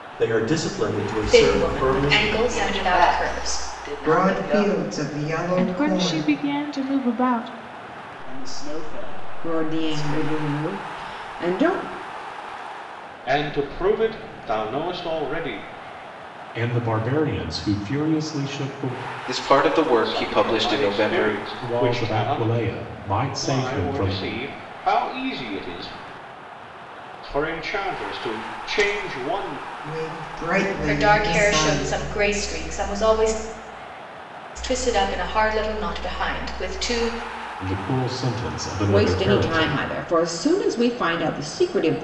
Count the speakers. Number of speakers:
10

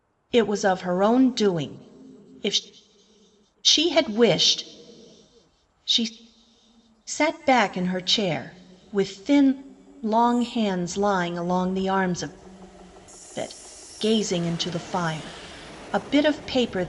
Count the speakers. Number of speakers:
1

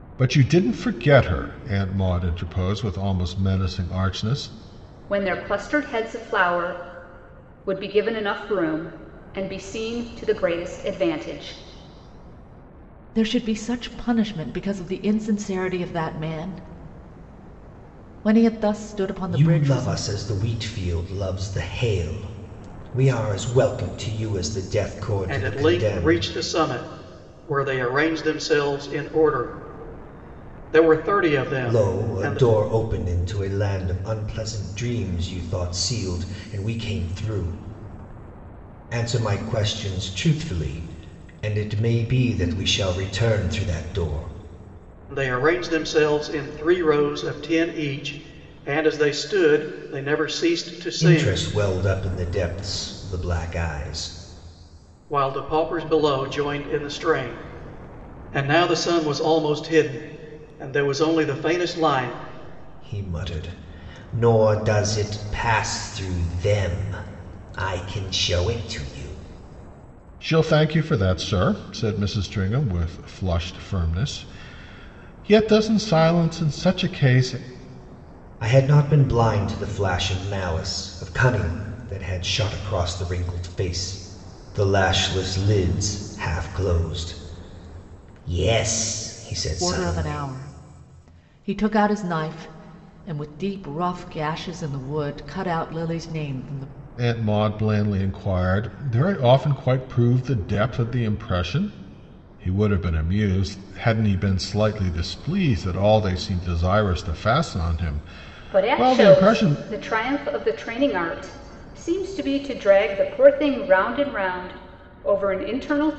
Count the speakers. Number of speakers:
5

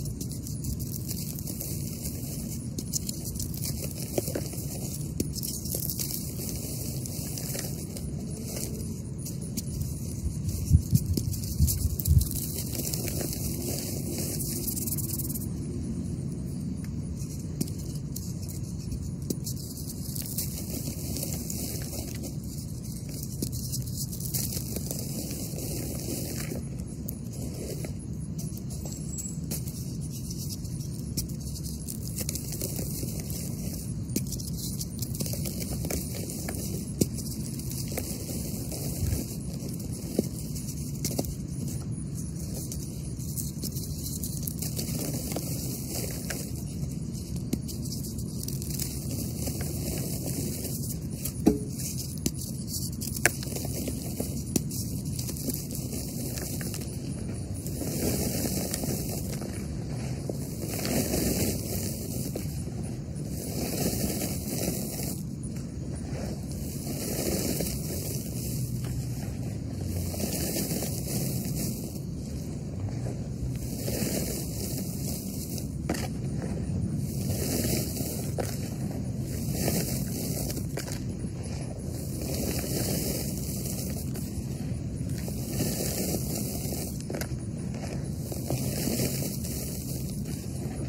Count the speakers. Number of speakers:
0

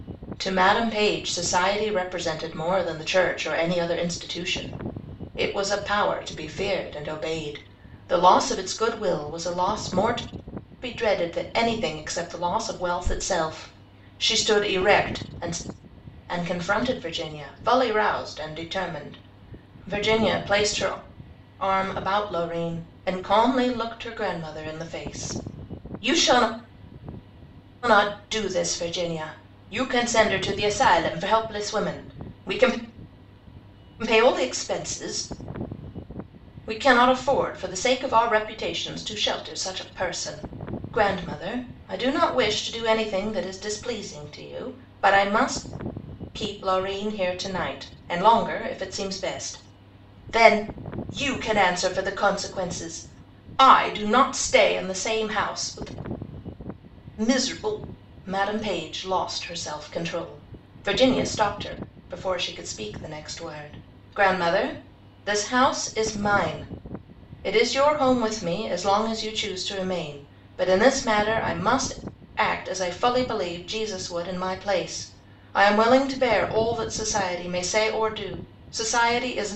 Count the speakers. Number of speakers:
1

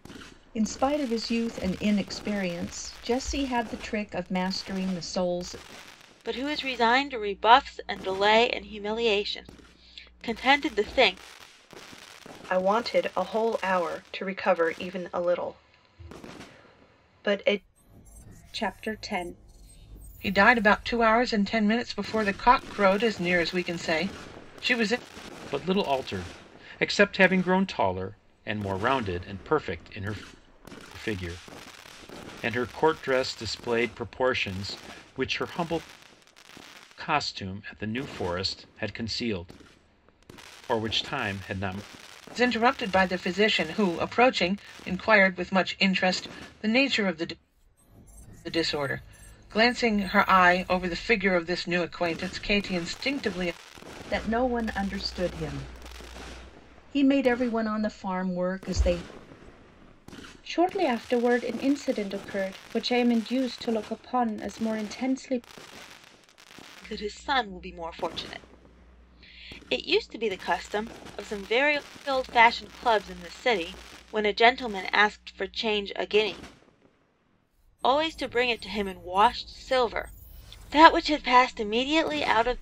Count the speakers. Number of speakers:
6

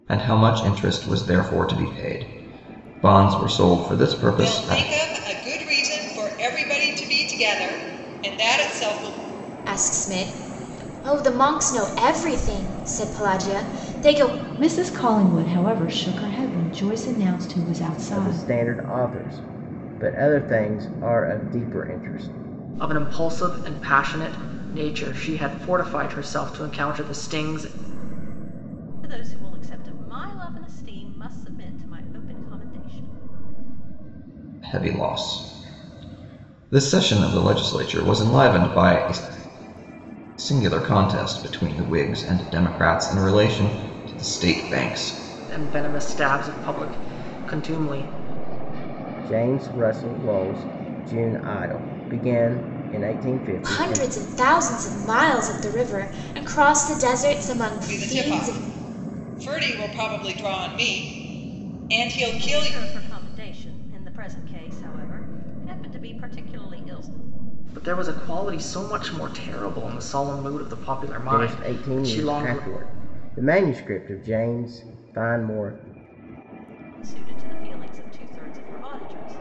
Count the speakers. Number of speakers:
7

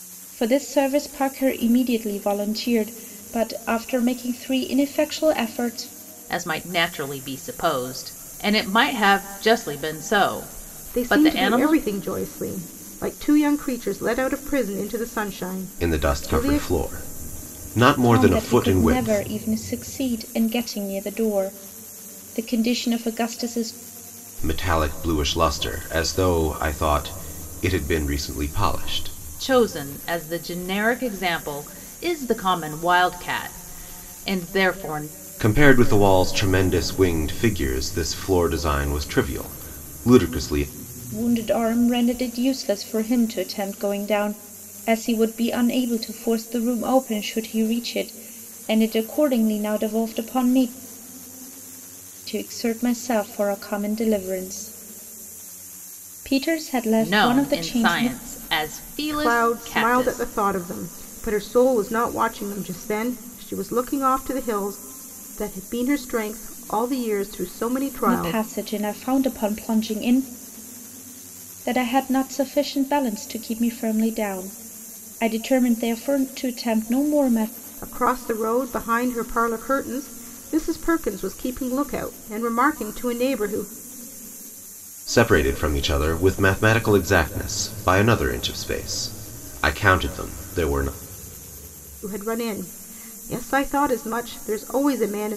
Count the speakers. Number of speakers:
4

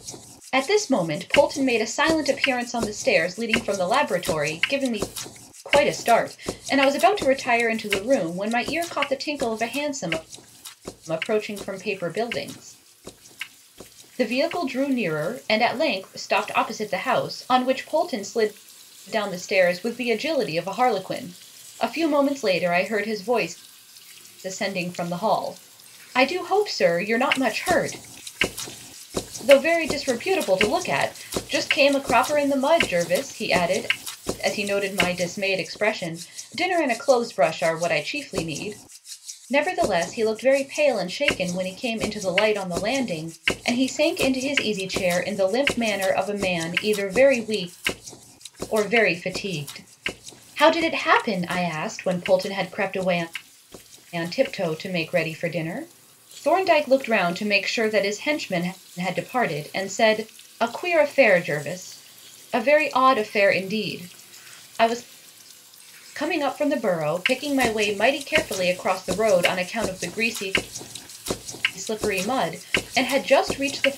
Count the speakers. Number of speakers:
1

